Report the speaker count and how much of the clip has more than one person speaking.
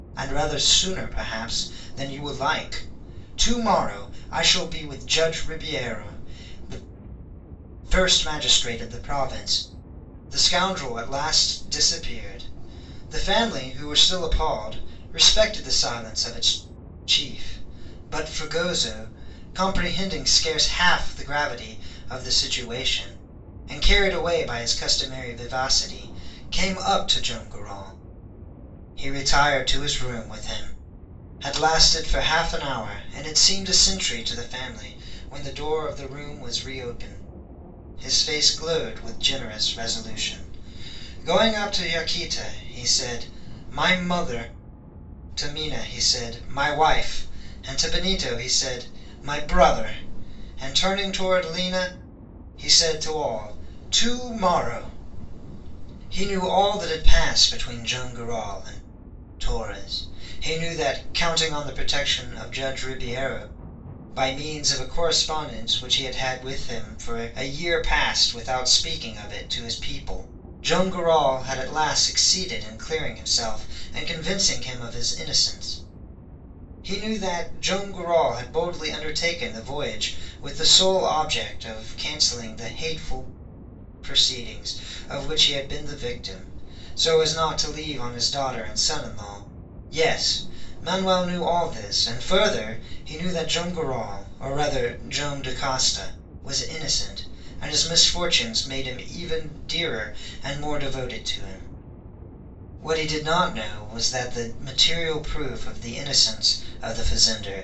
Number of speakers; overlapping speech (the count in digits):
1, no overlap